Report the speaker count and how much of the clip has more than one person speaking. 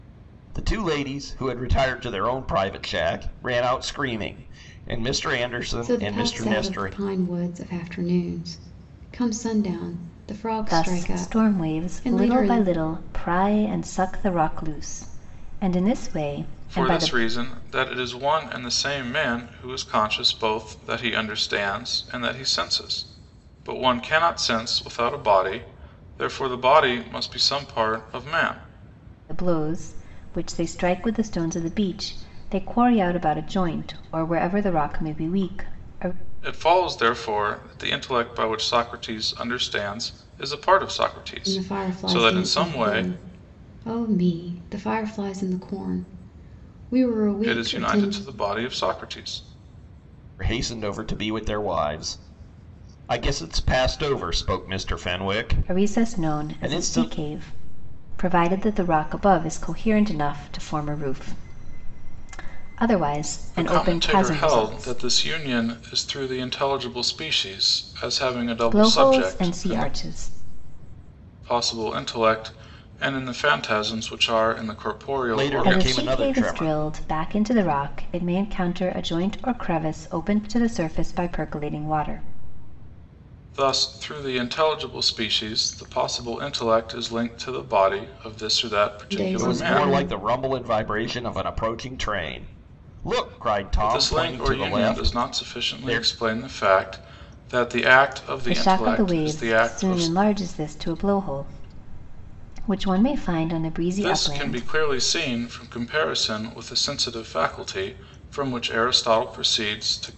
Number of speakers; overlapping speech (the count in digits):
4, about 16%